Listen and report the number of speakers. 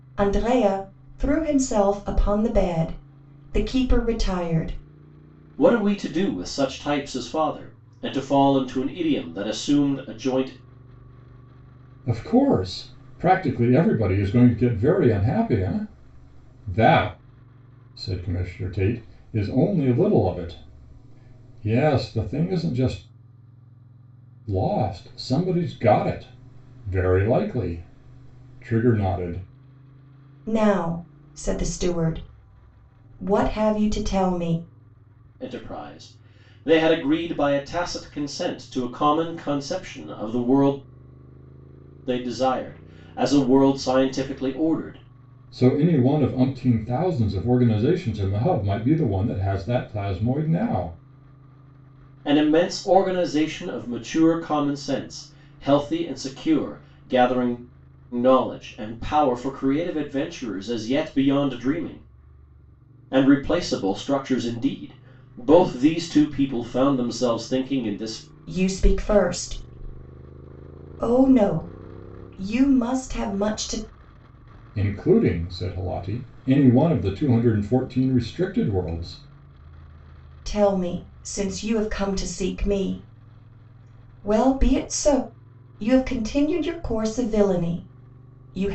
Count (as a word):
three